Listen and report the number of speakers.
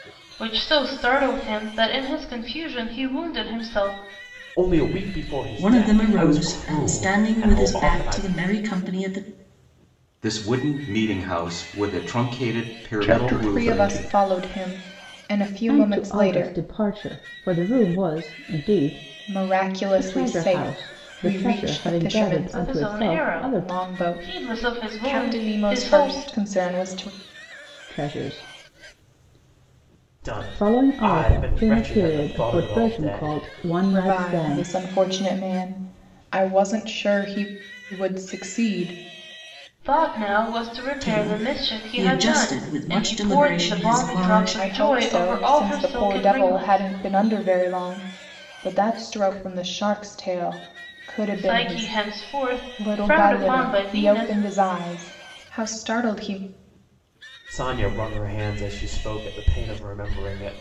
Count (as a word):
seven